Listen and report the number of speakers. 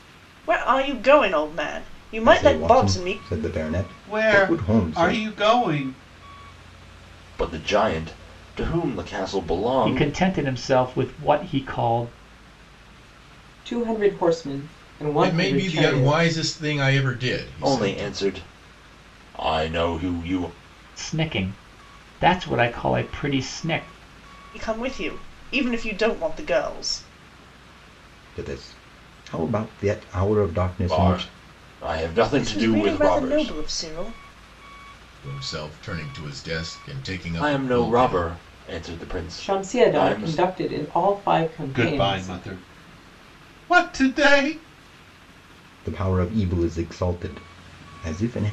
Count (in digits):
7